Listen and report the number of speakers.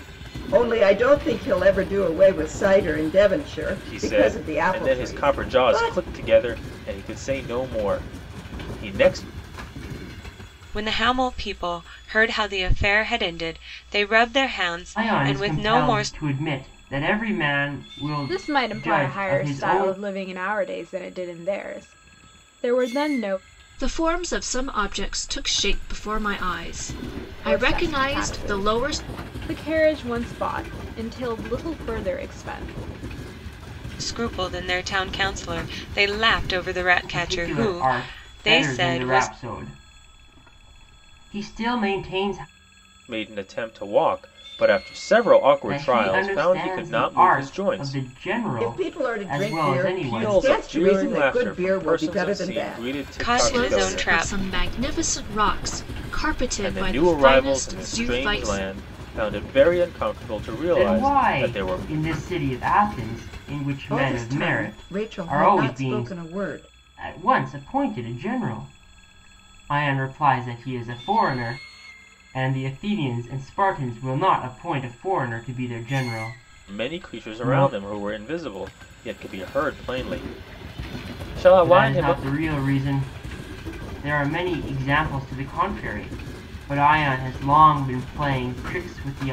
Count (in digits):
6